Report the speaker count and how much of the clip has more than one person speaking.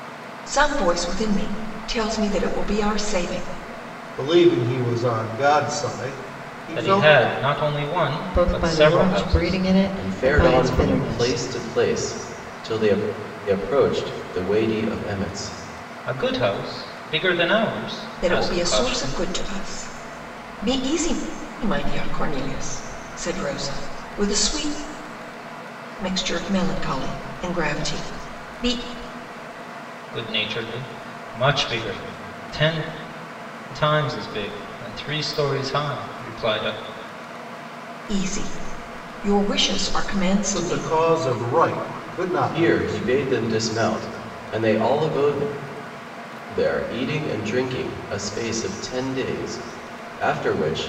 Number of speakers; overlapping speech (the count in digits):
5, about 10%